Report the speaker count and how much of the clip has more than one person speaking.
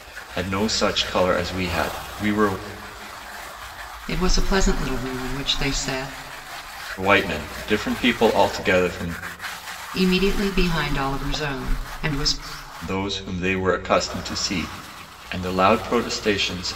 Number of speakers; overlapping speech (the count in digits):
2, no overlap